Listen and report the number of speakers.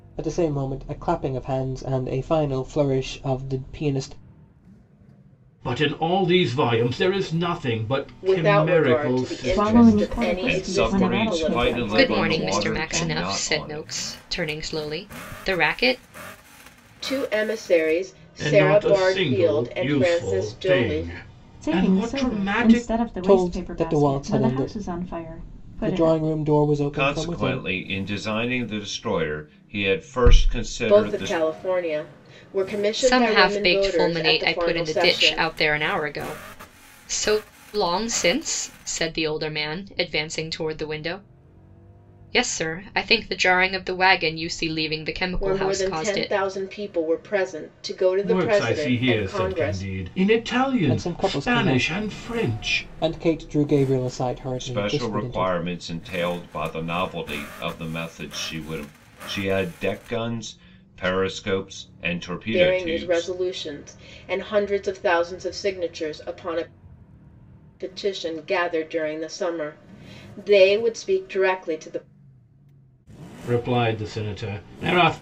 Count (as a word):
six